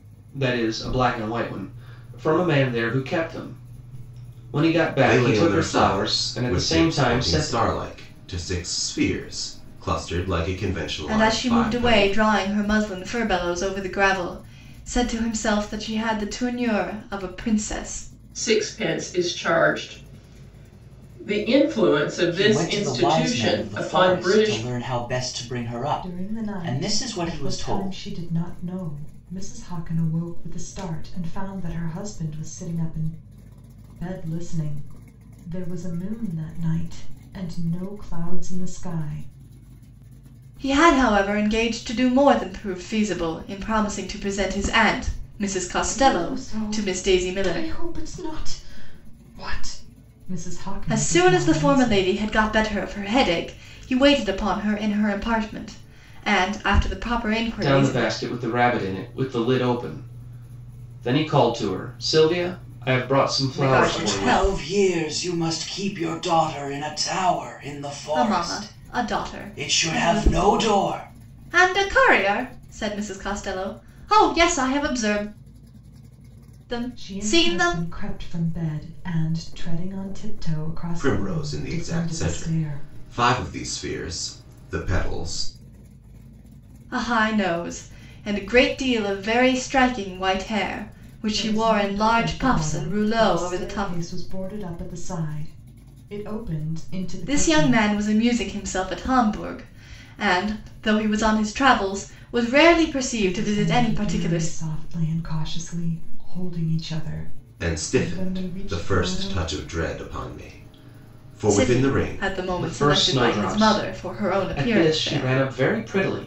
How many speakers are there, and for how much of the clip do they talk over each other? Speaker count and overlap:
6, about 25%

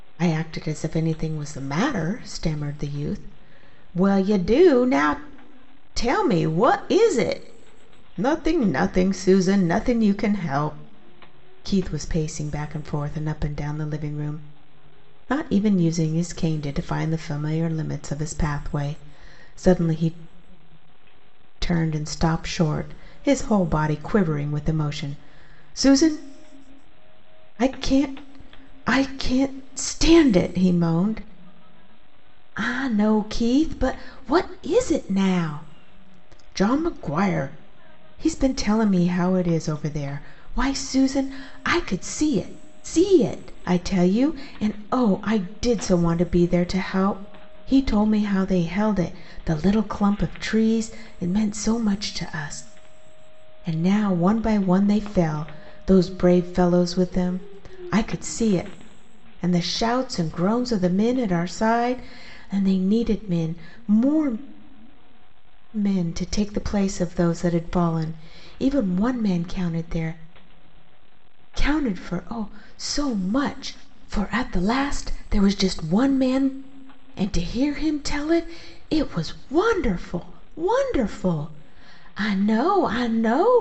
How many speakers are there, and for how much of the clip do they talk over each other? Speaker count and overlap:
1, no overlap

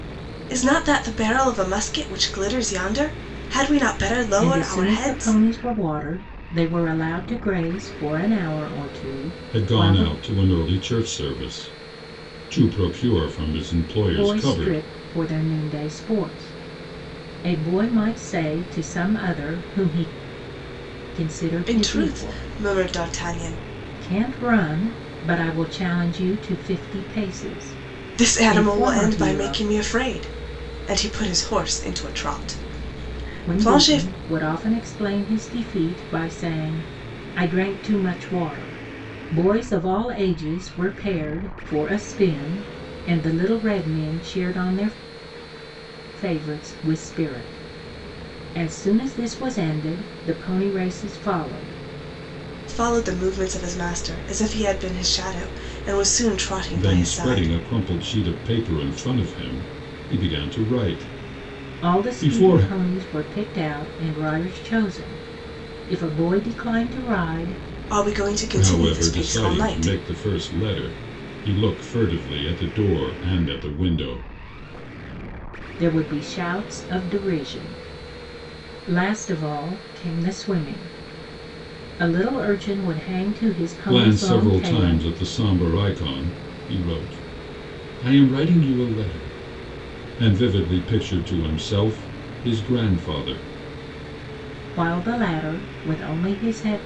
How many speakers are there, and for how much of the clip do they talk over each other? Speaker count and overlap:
3, about 10%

